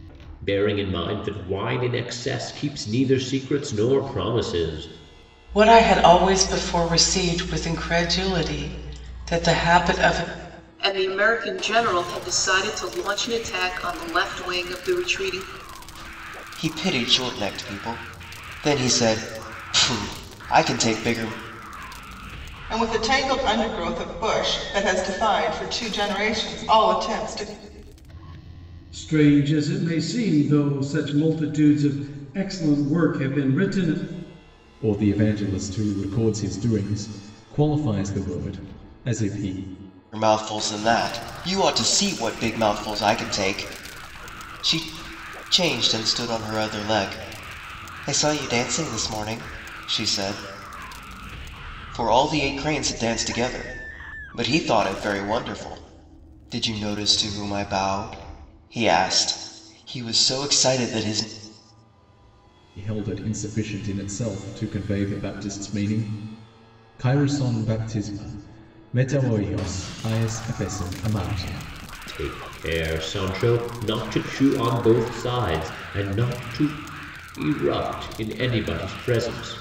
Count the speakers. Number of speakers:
seven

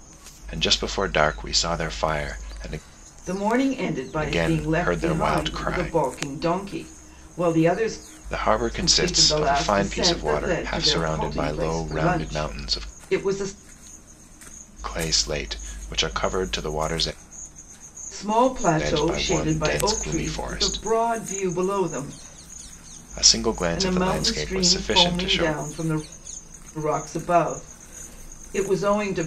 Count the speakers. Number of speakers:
two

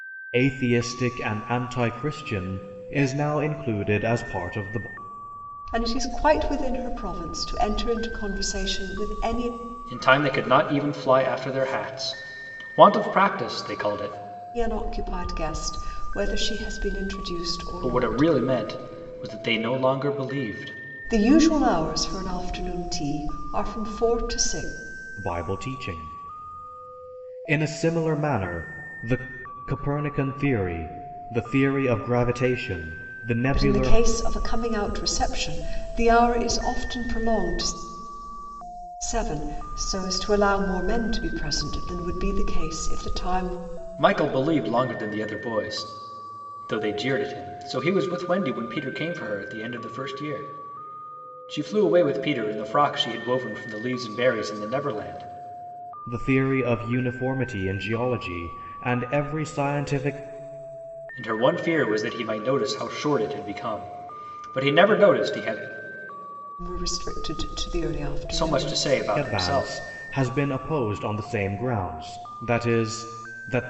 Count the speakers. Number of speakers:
three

